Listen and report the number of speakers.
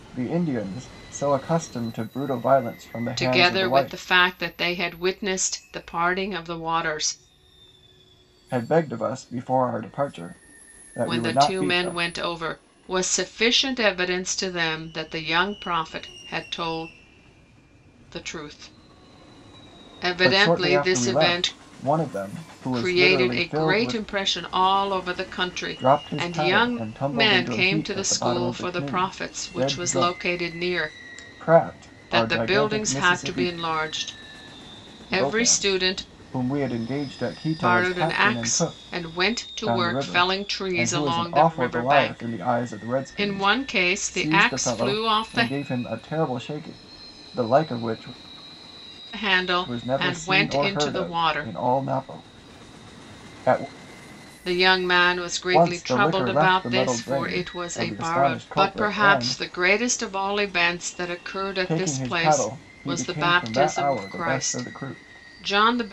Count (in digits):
2